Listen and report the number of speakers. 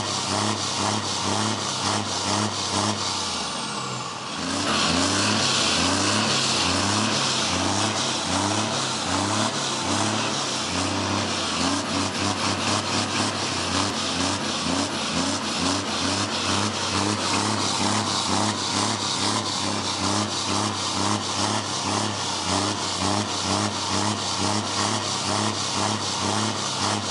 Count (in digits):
0